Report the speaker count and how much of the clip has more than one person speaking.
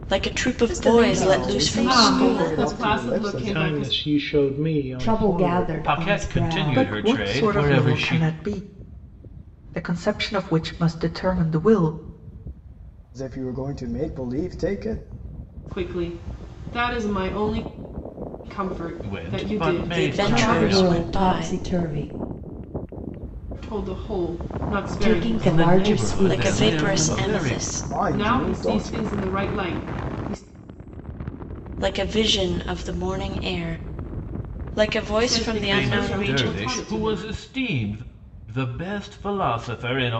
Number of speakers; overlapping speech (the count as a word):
eight, about 37%